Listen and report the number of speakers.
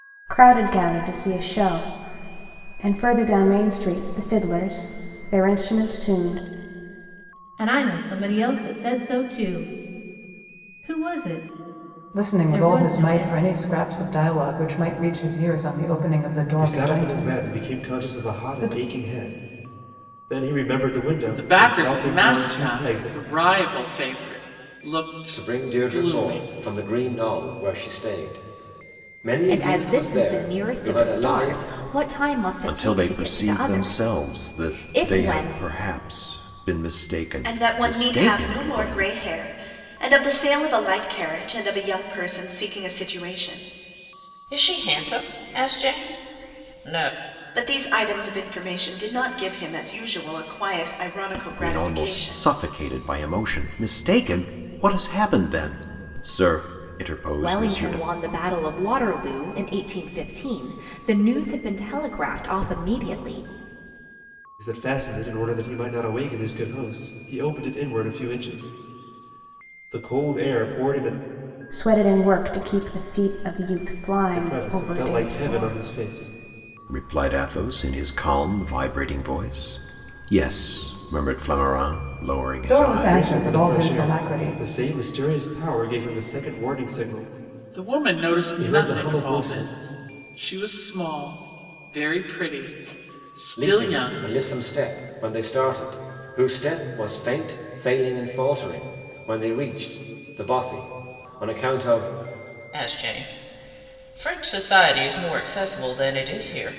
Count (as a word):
ten